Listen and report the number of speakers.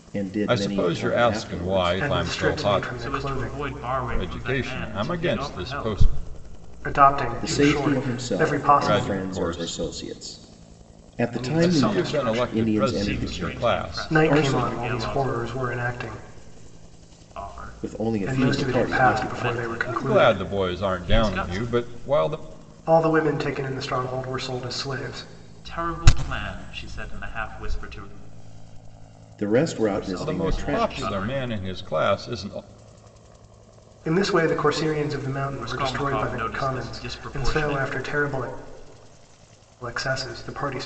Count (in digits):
4